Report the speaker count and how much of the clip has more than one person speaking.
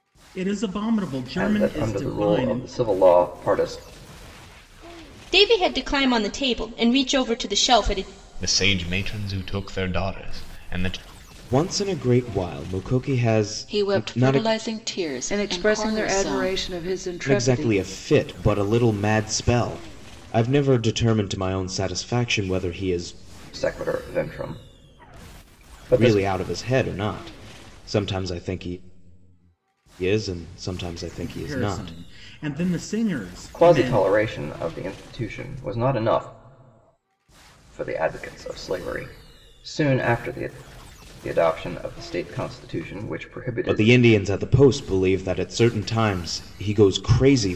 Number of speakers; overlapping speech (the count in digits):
7, about 12%